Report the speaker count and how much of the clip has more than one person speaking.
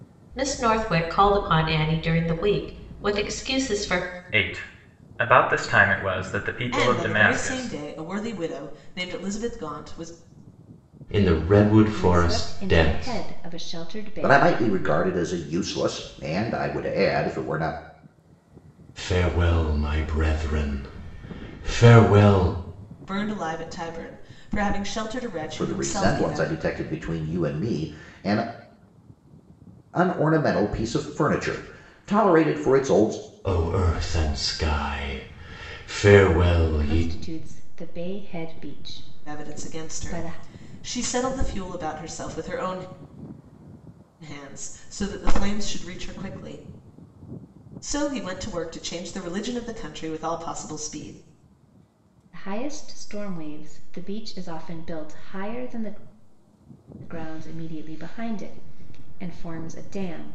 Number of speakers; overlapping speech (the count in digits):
6, about 9%